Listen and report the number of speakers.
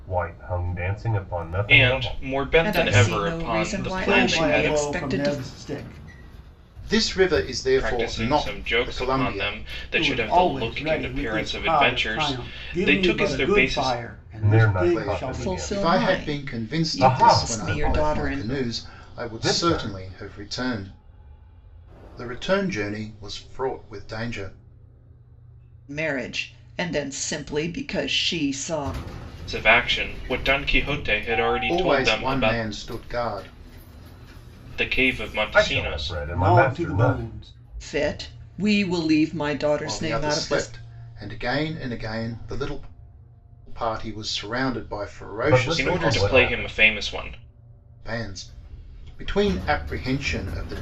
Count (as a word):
five